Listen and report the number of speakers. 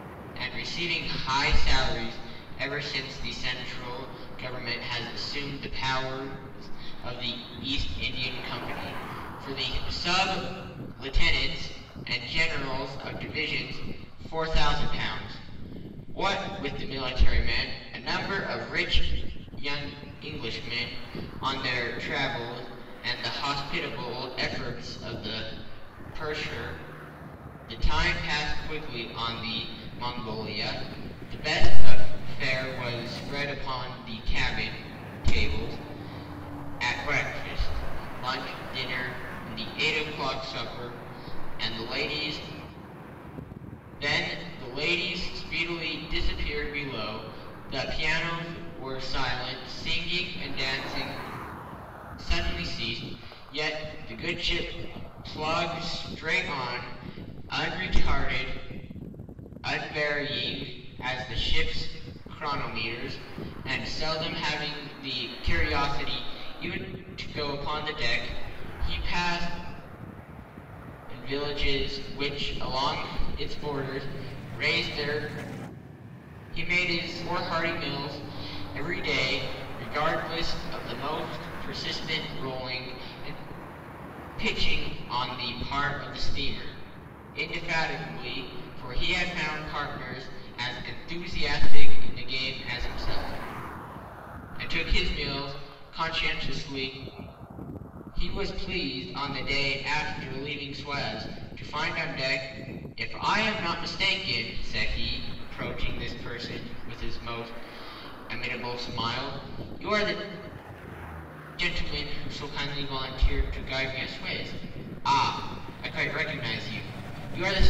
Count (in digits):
1